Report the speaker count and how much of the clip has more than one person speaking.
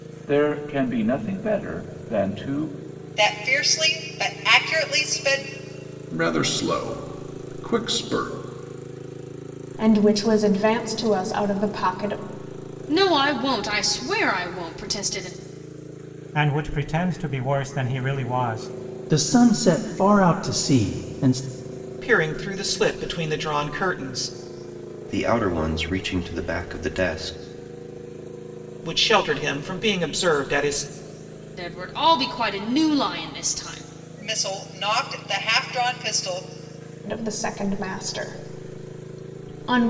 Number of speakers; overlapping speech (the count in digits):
9, no overlap